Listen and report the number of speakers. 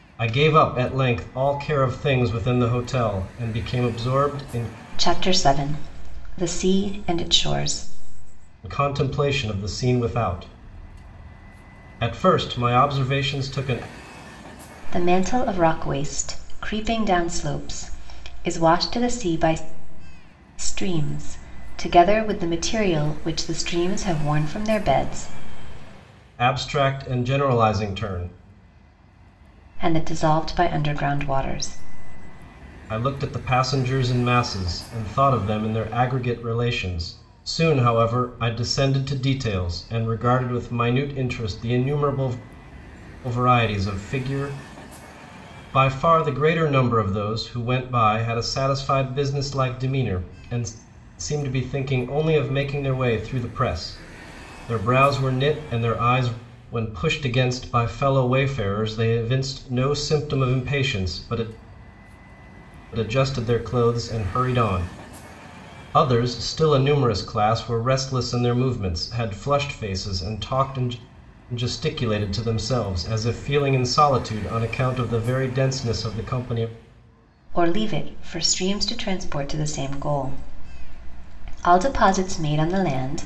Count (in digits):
2